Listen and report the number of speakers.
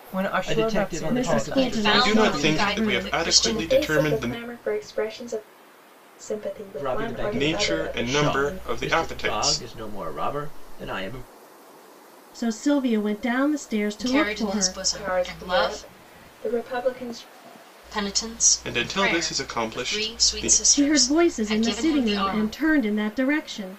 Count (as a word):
six